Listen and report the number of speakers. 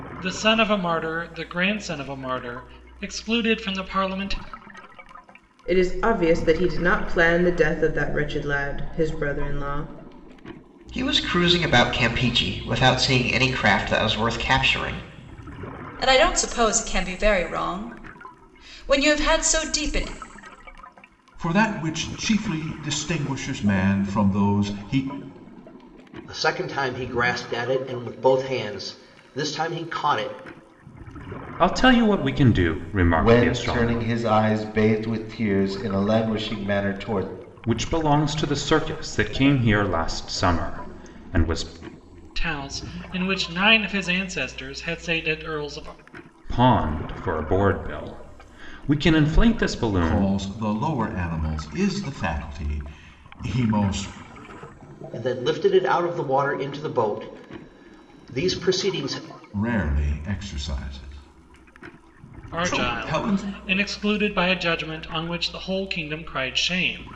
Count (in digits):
8